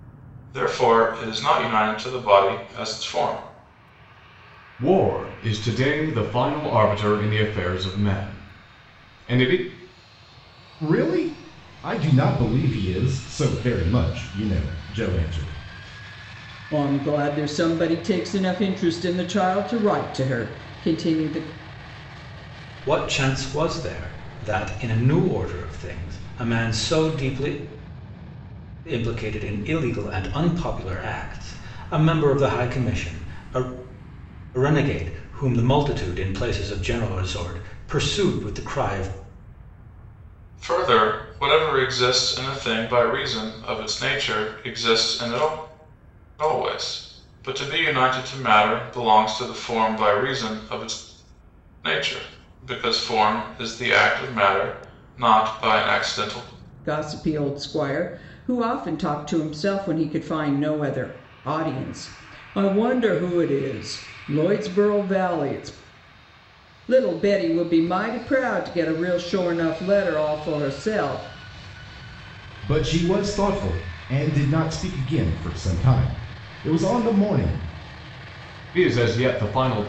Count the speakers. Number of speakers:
five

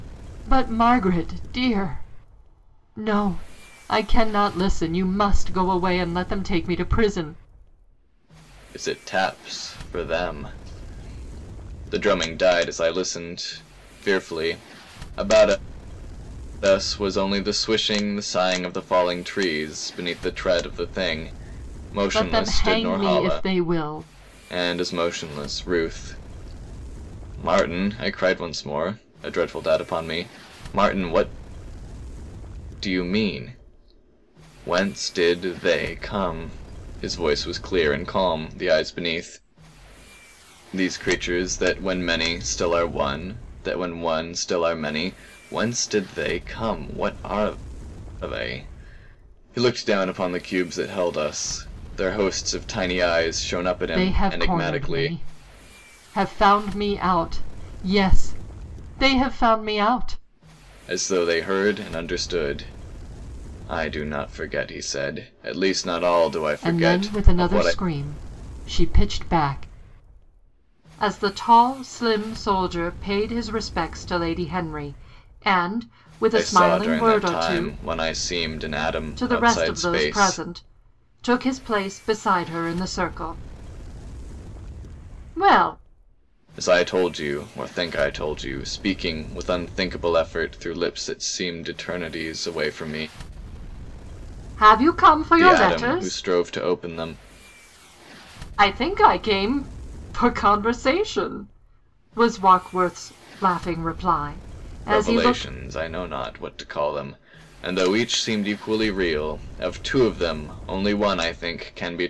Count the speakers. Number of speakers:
two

